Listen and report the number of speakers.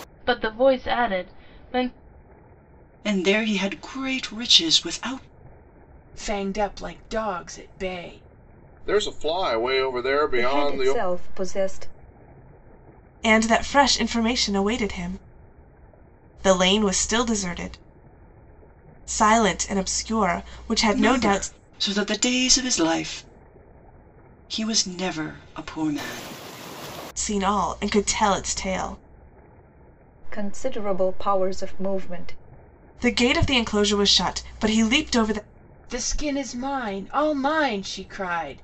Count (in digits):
6